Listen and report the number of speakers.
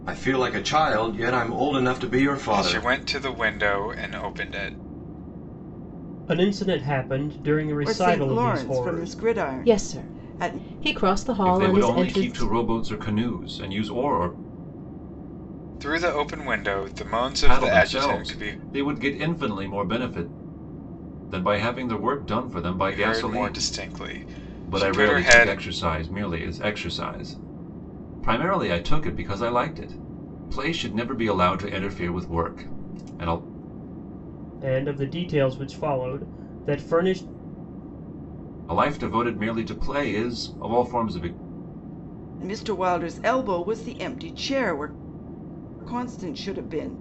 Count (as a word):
six